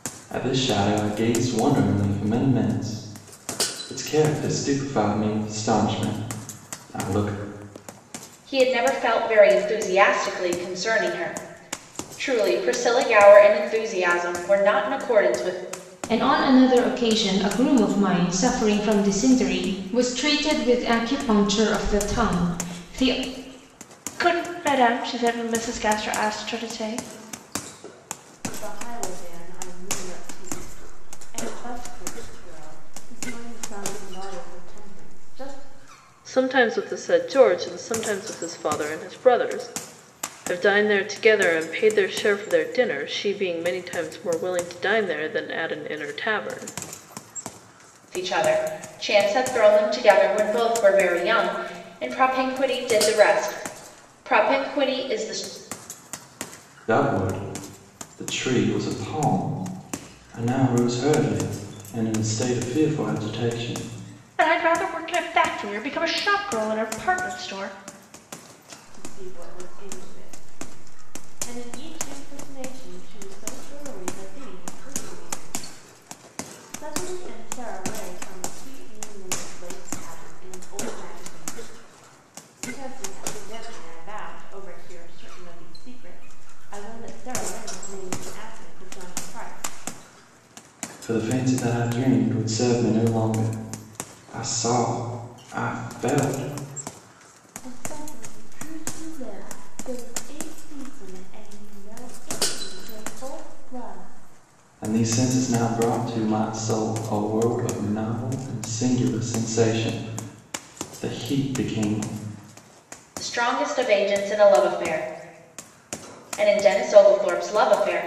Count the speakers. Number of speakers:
6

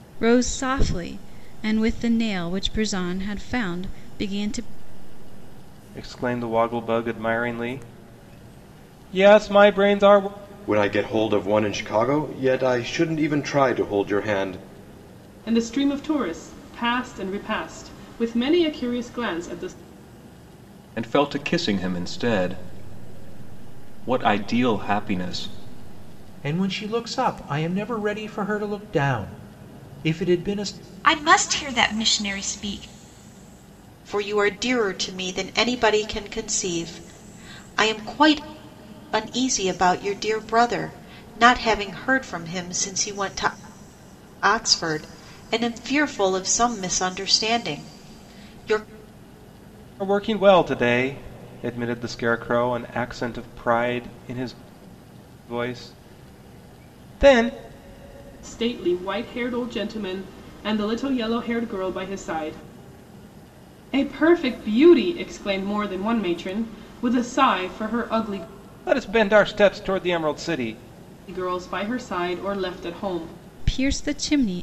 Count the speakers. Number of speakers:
8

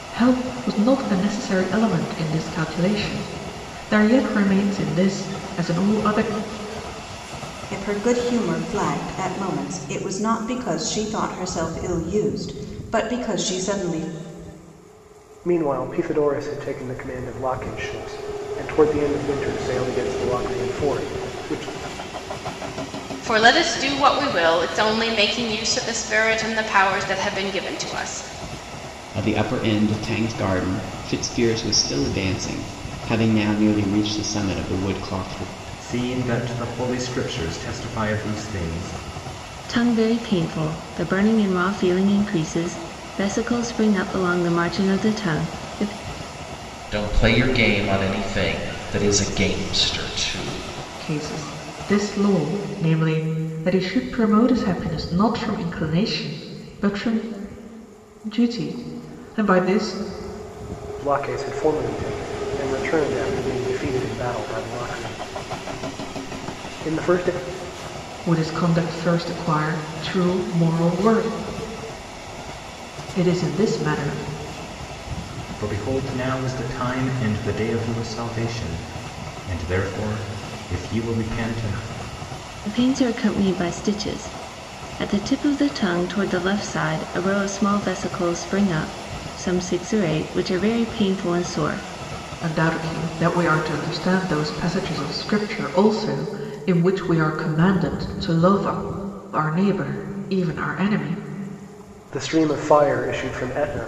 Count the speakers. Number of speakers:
8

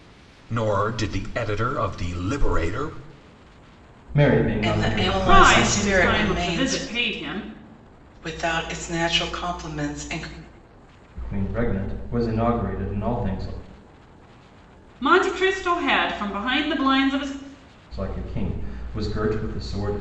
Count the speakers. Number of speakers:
4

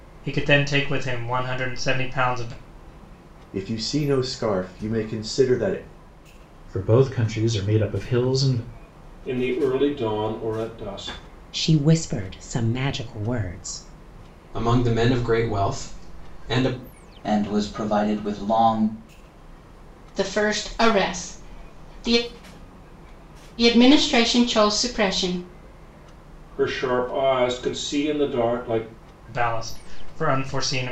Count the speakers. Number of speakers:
8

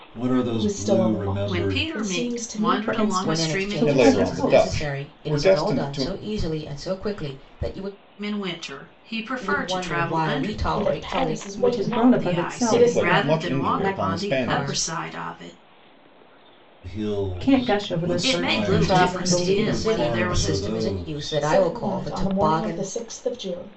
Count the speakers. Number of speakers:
6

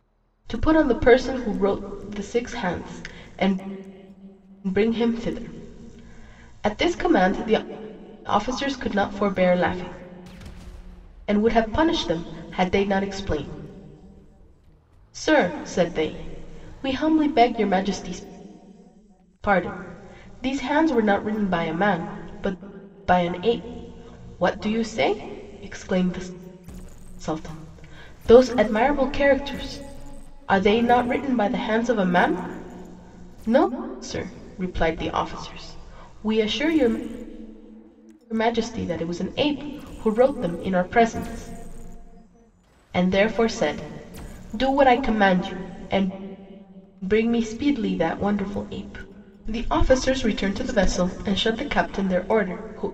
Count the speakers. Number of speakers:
1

